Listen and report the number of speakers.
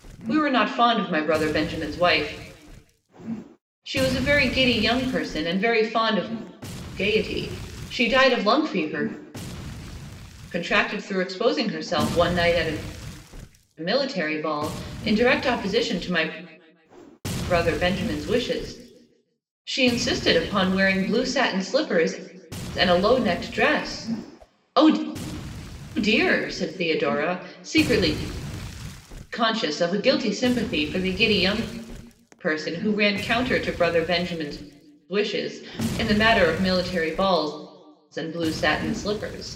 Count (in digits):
1